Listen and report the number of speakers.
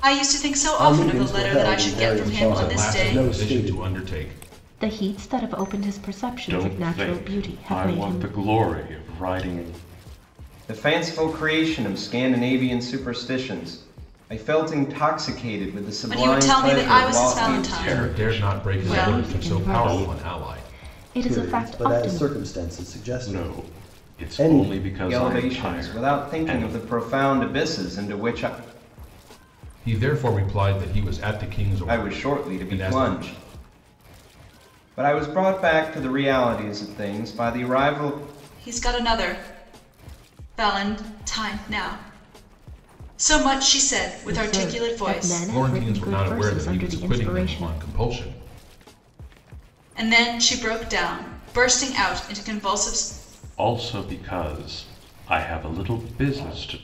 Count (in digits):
6